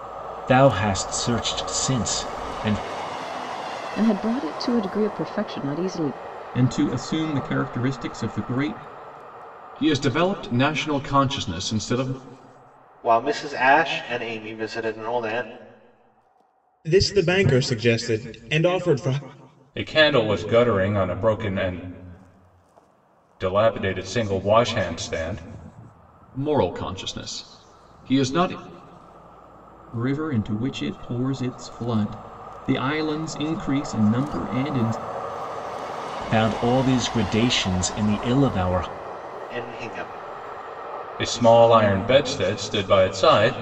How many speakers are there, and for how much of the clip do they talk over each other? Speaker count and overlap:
7, no overlap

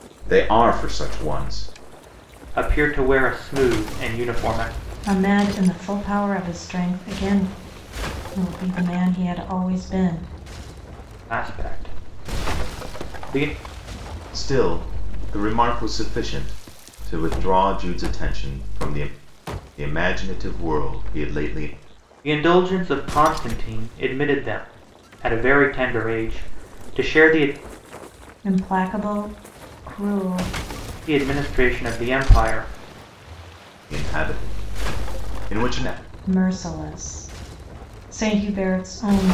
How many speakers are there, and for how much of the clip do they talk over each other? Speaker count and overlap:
3, no overlap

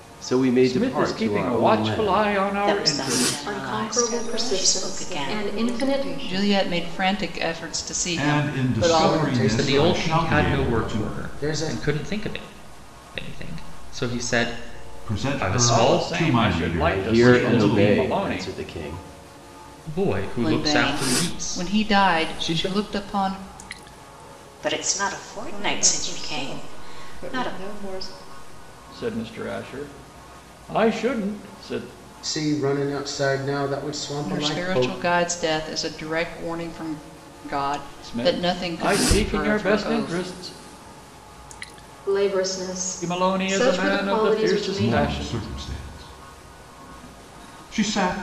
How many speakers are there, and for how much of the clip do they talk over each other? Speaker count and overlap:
9, about 48%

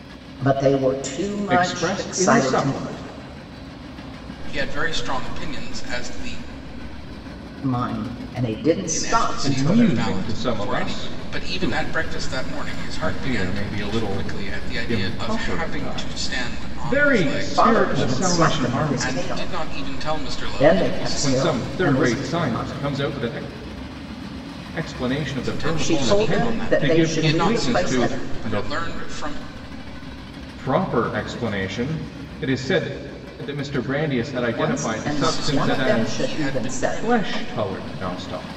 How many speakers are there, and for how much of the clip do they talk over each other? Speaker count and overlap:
3, about 47%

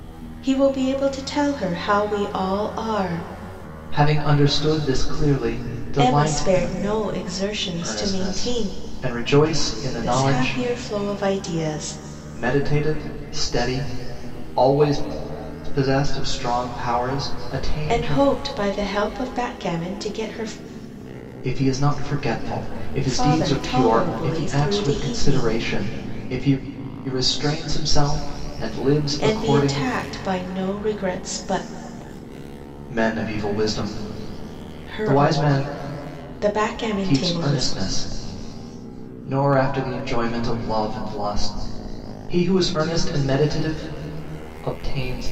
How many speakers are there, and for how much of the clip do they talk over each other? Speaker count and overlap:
2, about 16%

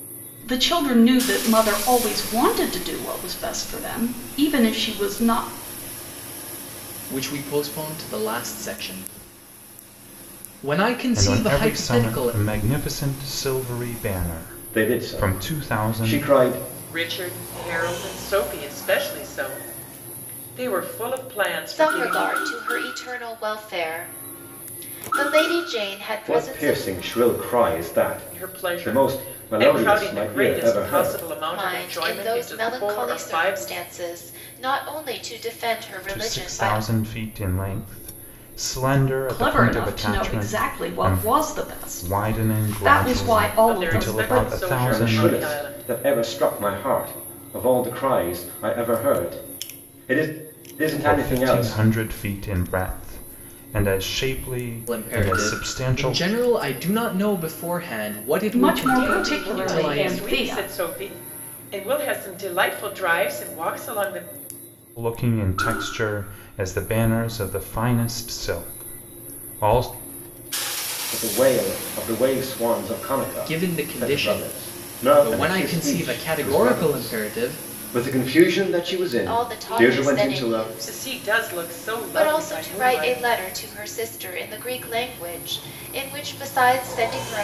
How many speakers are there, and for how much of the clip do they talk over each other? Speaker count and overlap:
6, about 31%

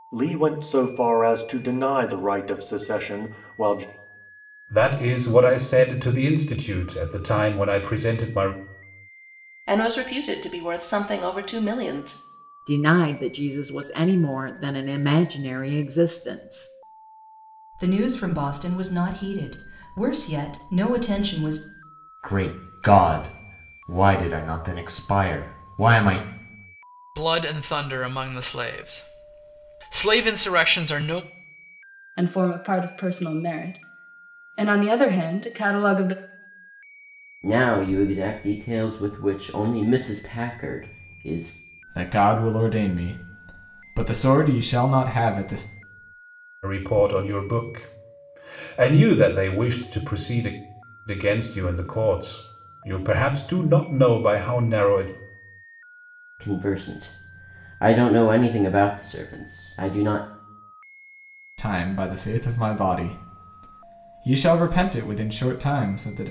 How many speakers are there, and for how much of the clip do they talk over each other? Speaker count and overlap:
10, no overlap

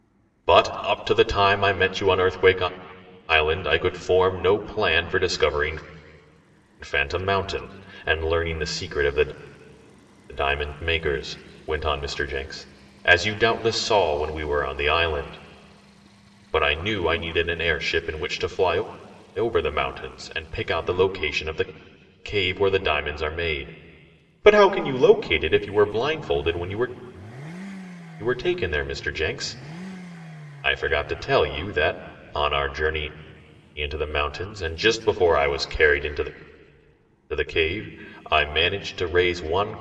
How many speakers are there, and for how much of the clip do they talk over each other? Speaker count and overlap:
1, no overlap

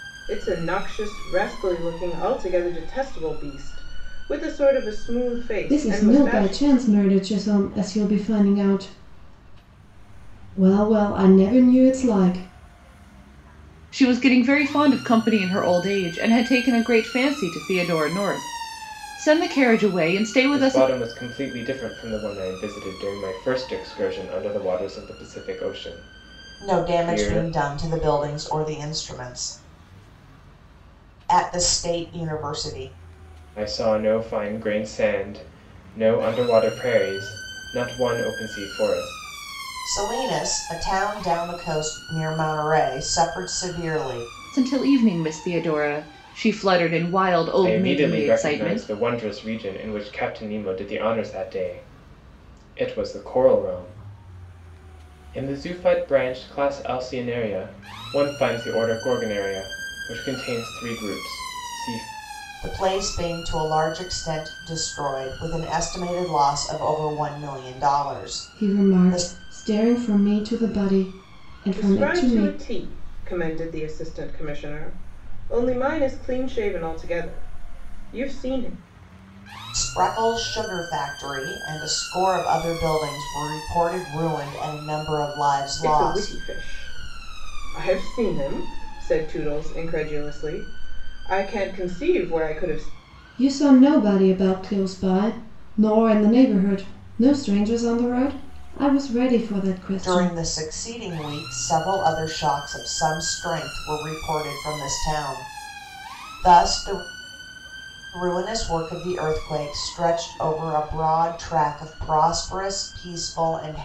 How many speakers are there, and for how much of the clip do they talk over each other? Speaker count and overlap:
5, about 6%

